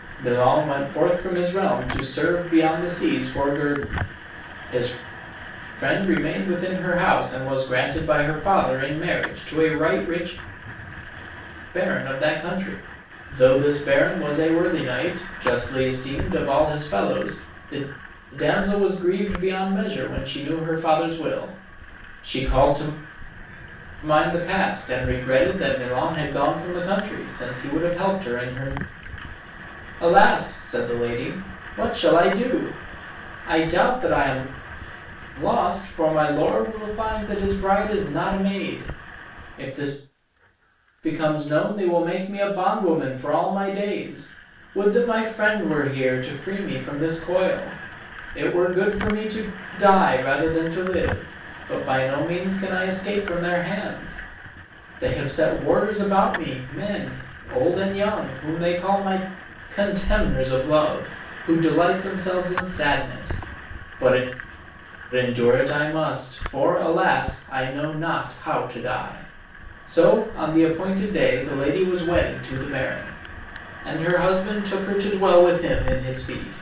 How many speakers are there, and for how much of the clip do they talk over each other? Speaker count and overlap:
1, no overlap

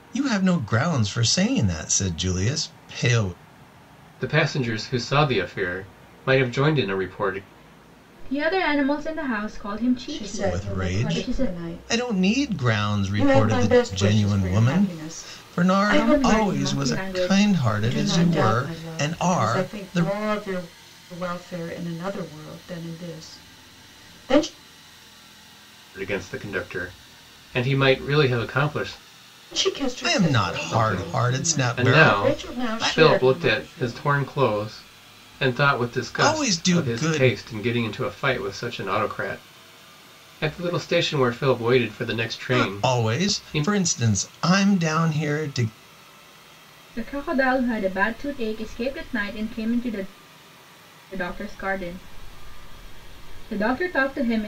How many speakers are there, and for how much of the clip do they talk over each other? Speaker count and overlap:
4, about 28%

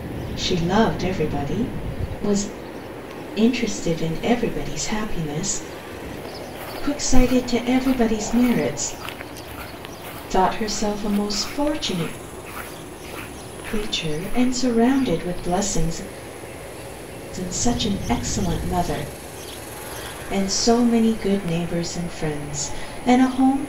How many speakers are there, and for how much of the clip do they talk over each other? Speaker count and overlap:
1, no overlap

